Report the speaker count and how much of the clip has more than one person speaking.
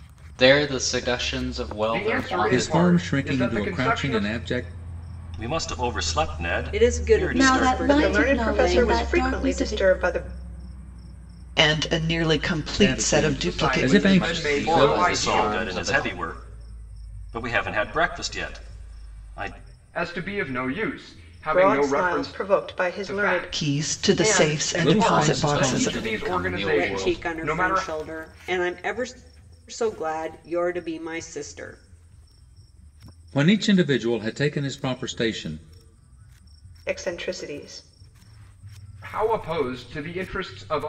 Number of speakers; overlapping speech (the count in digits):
8, about 36%